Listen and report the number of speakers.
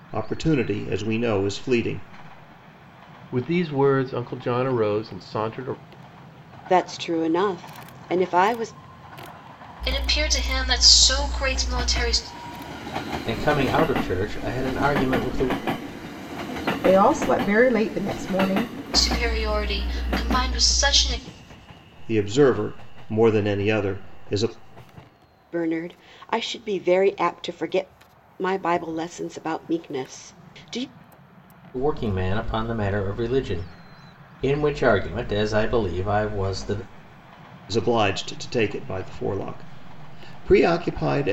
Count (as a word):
six